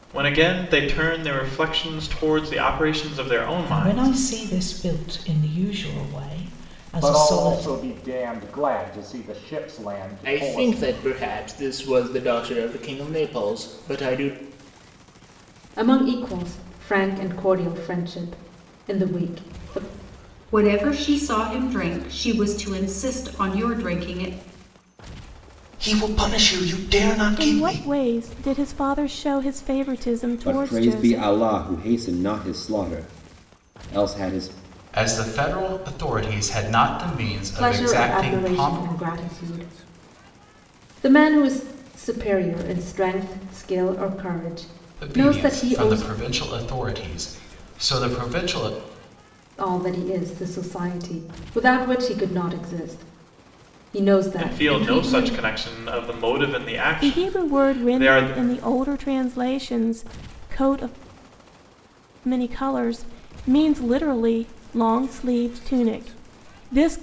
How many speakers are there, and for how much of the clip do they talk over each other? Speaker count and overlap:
10, about 13%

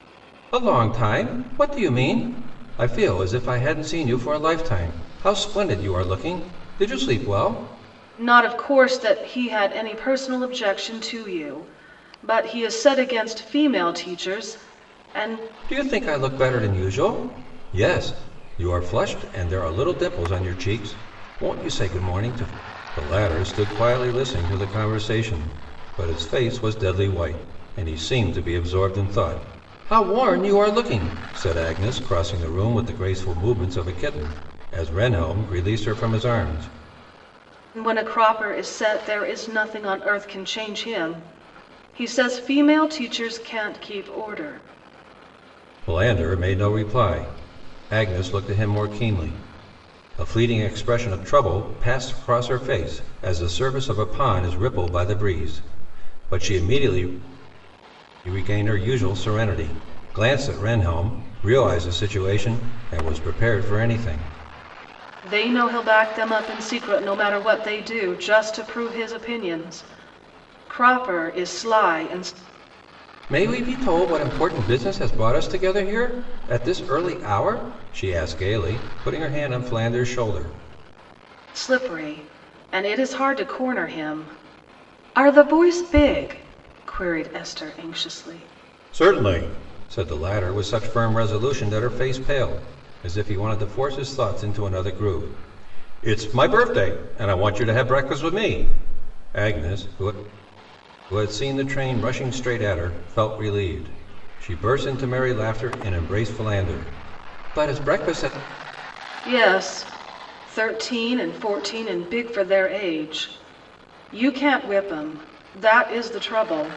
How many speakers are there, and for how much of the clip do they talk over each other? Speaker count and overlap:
2, no overlap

